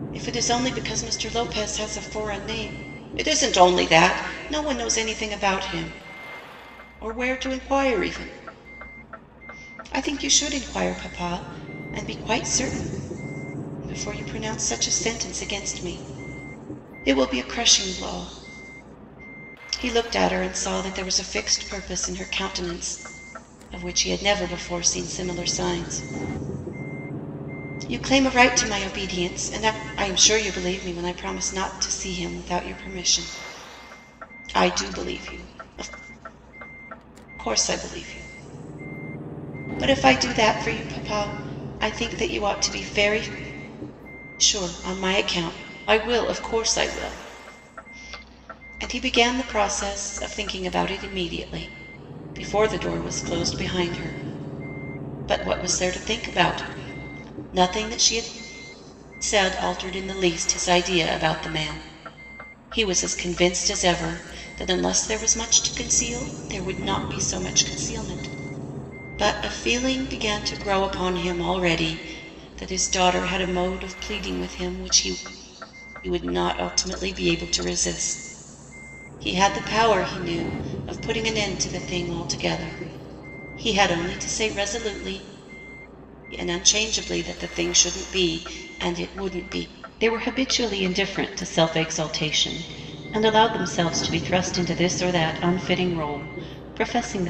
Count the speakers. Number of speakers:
one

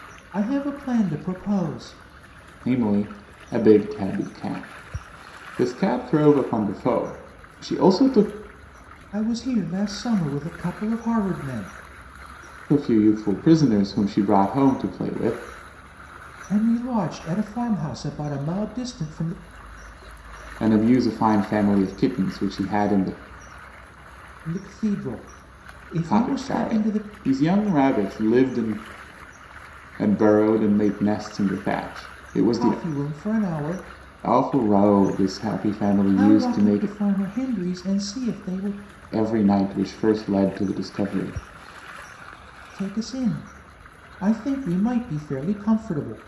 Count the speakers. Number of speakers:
two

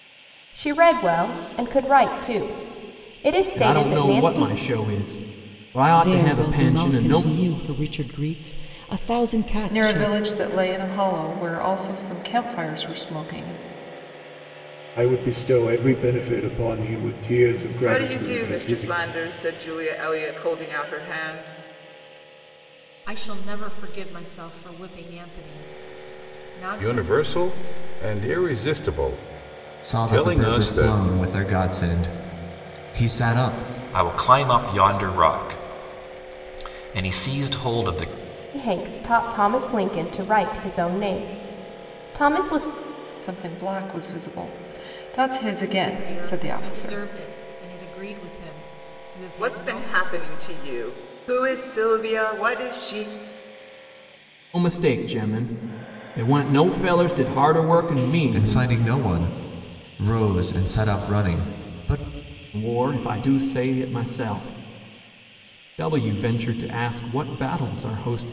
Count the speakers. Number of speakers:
ten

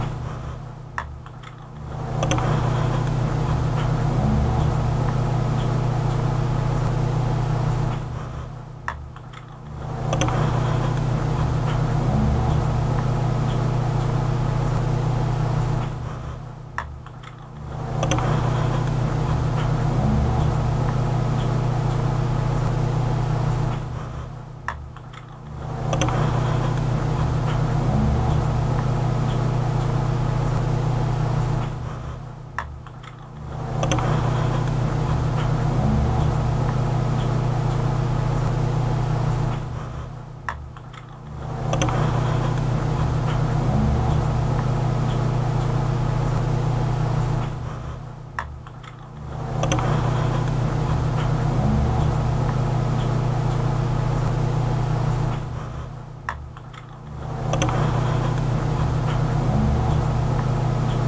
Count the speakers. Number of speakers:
zero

